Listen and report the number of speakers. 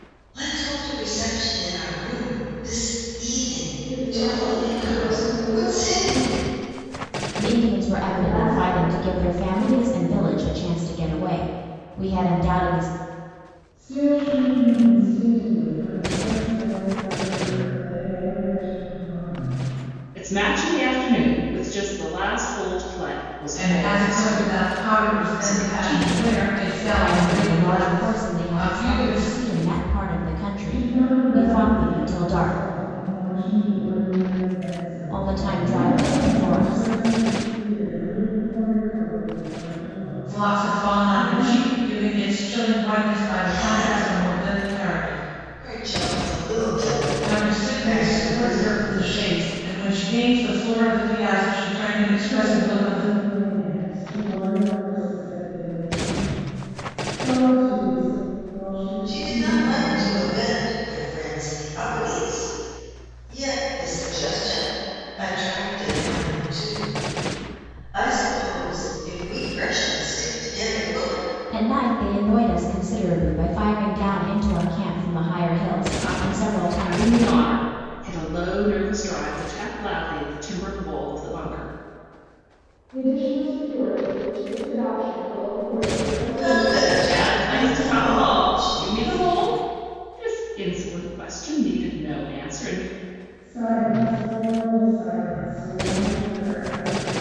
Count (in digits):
6